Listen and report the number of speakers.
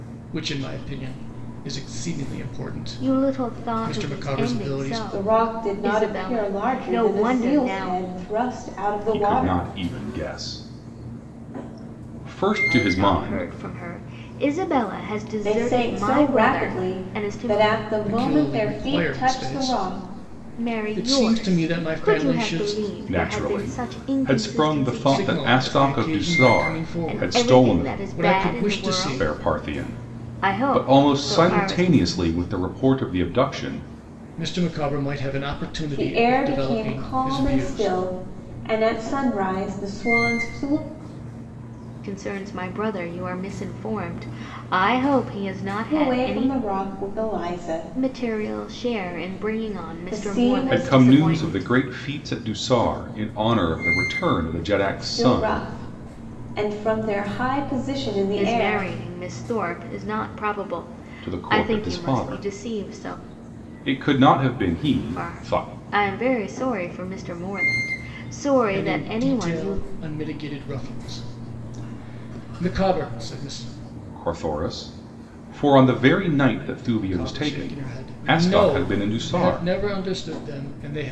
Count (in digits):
4